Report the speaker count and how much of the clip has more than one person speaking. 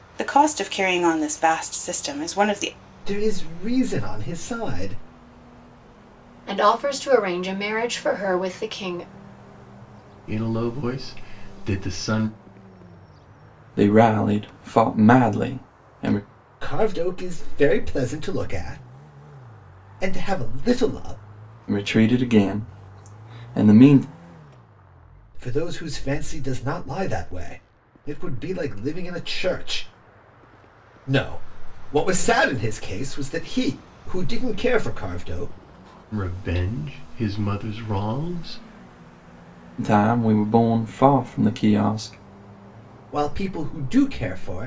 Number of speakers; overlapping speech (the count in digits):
5, no overlap